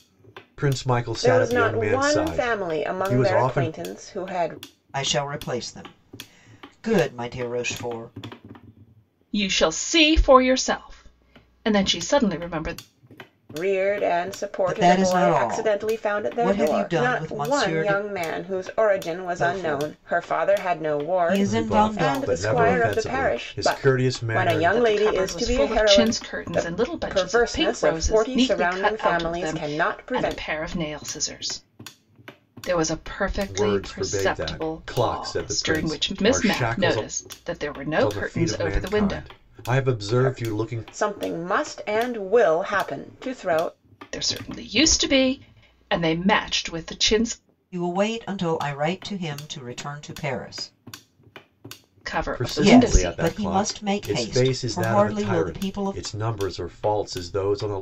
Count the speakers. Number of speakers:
four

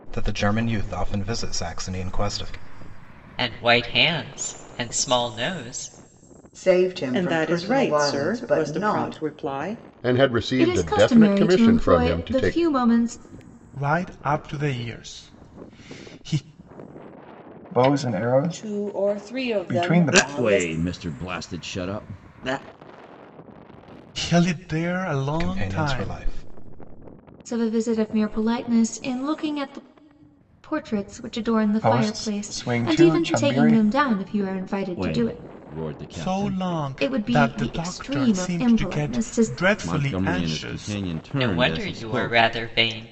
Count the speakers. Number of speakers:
ten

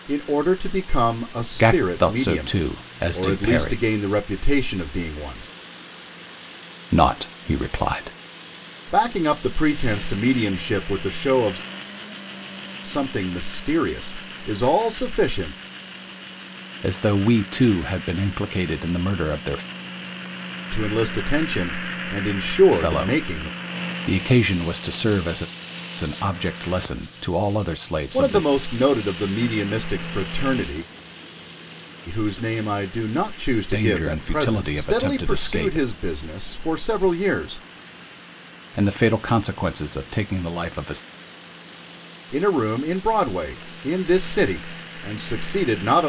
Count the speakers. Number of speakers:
two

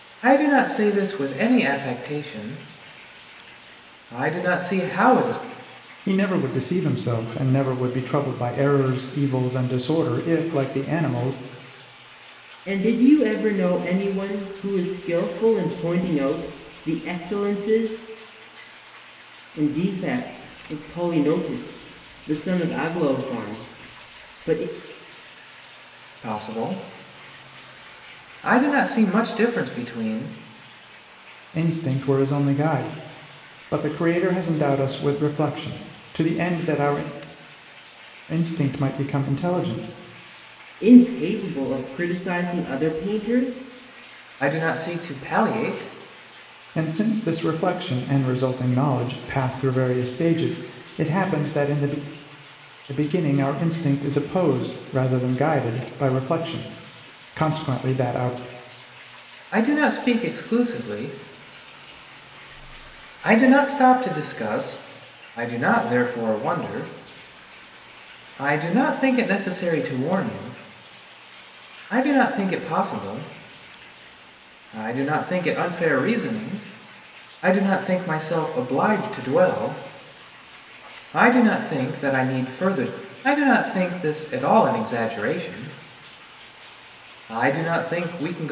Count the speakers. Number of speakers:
three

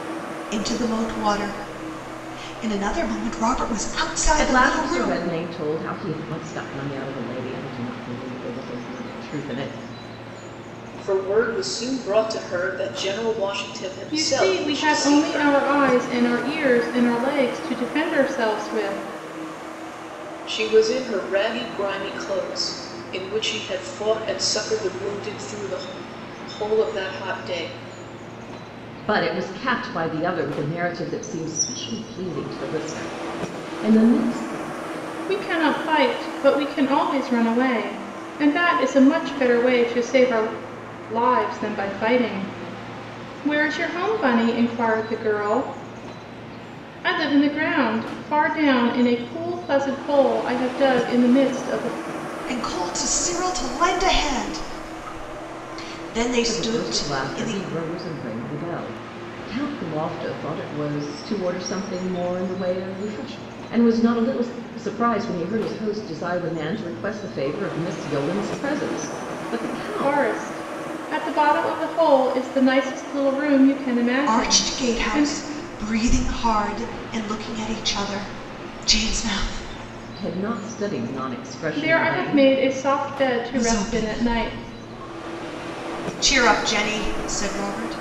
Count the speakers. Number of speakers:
four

